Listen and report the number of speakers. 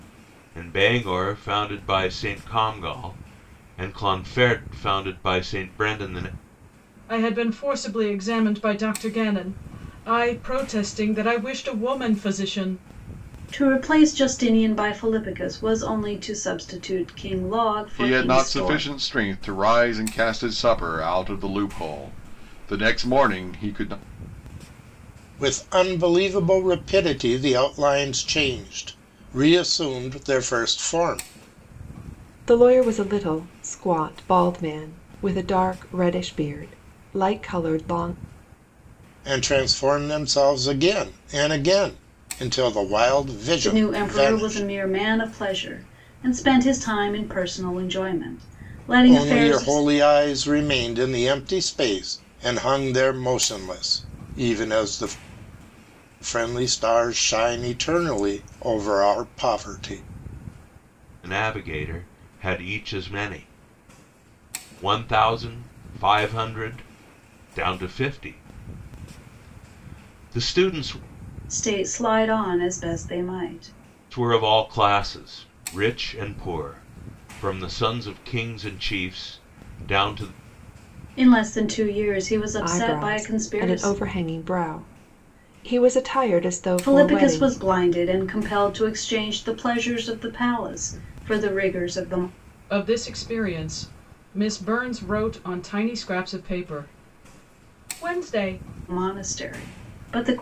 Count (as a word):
six